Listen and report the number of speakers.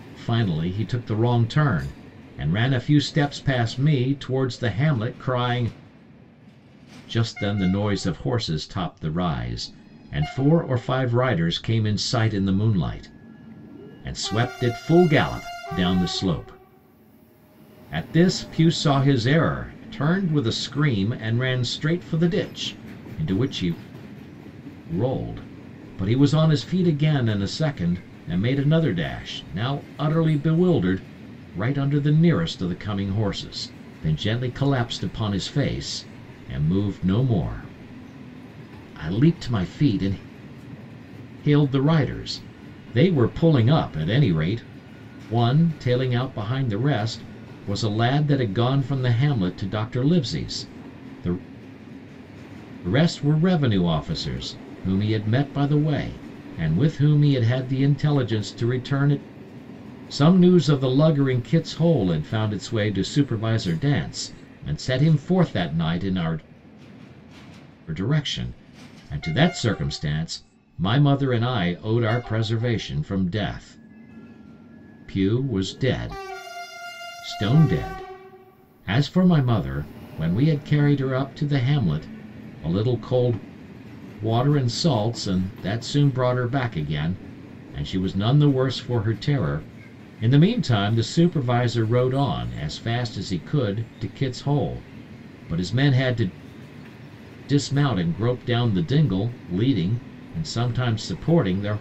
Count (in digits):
1